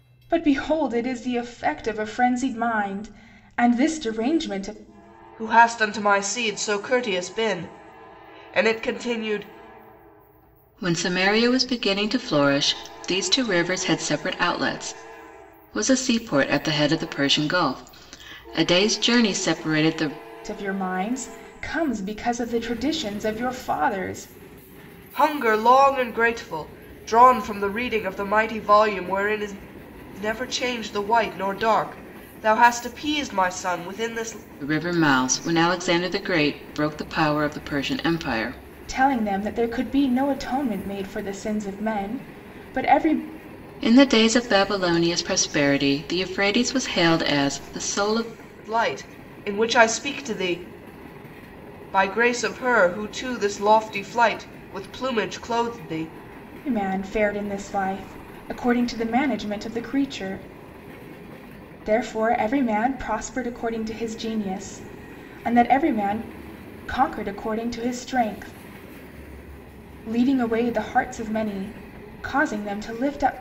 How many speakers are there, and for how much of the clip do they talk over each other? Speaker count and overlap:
three, no overlap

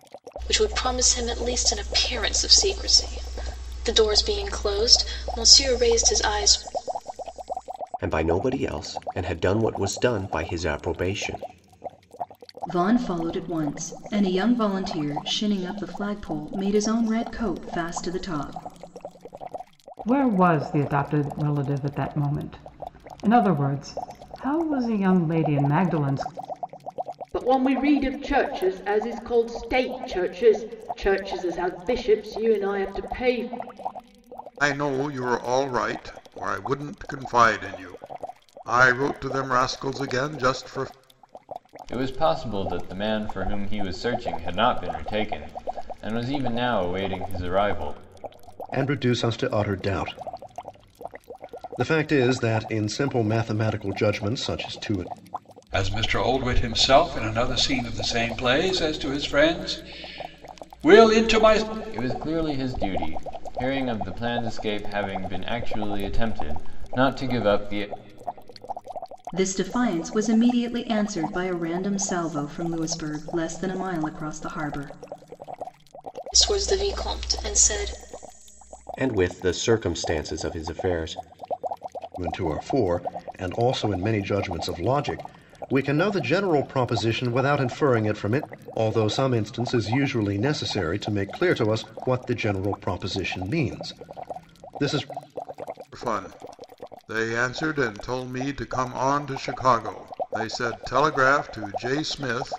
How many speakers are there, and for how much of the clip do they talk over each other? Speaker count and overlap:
nine, no overlap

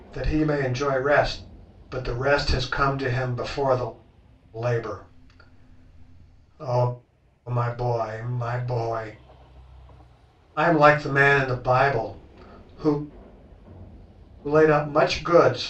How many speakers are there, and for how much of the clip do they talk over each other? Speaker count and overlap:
one, no overlap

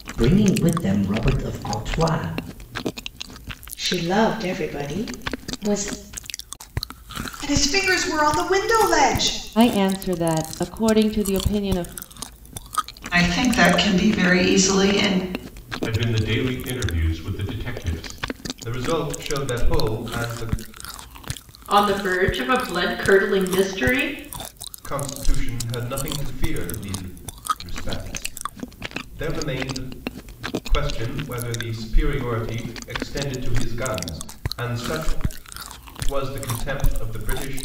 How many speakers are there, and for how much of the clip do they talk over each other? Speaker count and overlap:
eight, no overlap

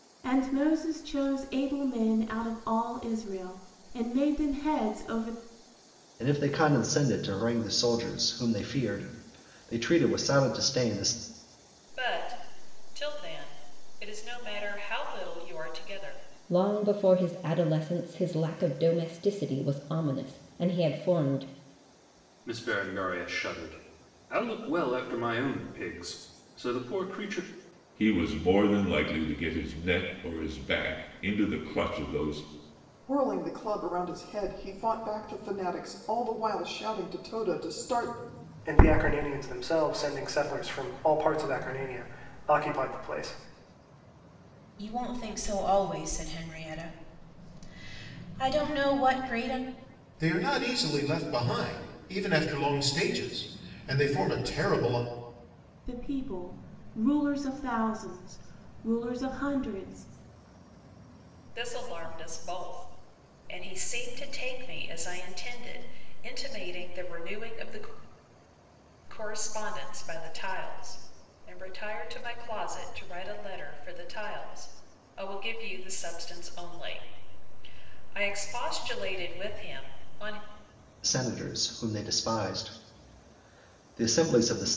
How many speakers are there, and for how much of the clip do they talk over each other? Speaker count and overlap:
ten, no overlap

